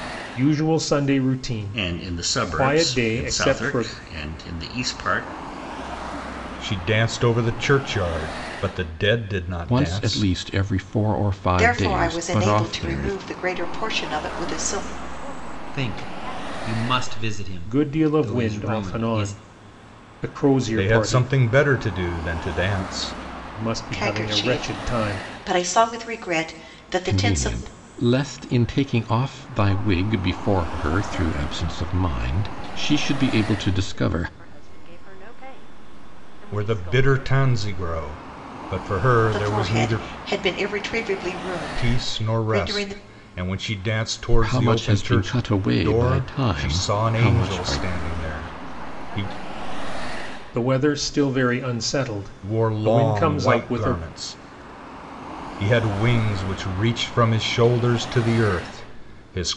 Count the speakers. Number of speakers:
seven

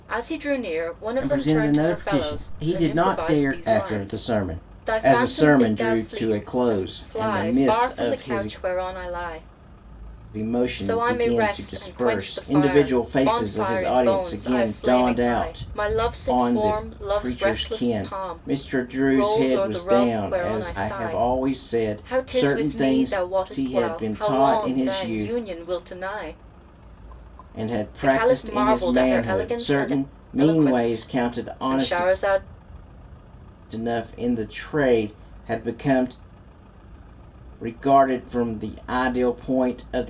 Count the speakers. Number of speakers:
two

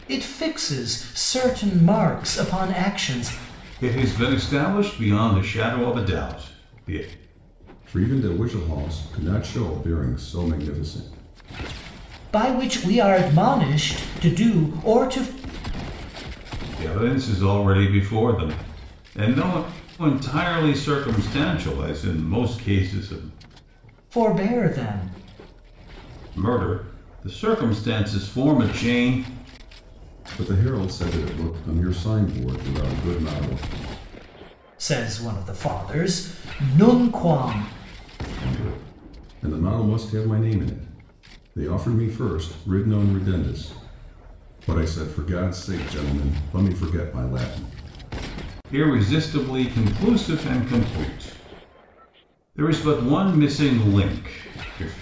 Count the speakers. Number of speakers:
three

